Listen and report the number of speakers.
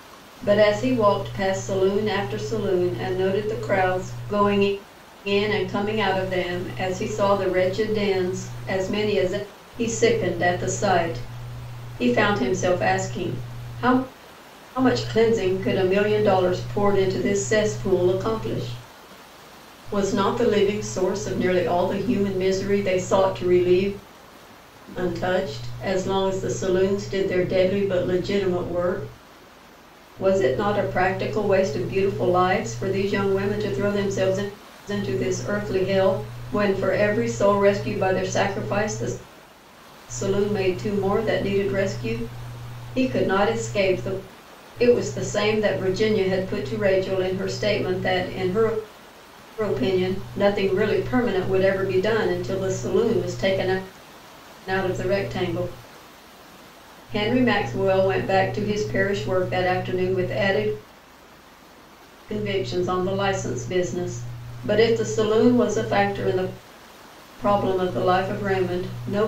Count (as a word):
one